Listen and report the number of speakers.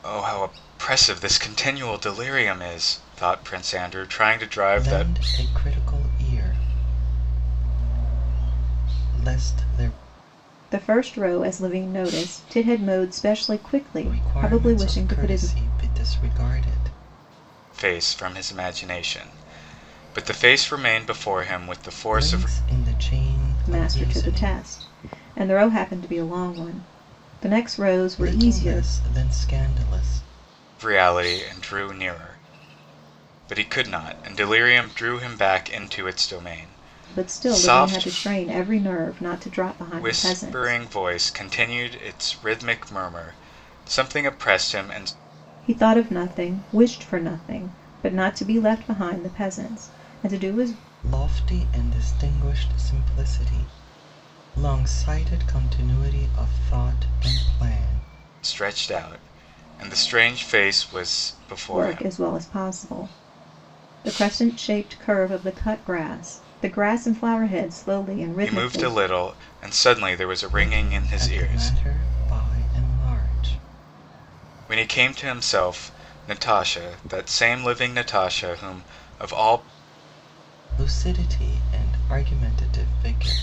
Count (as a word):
three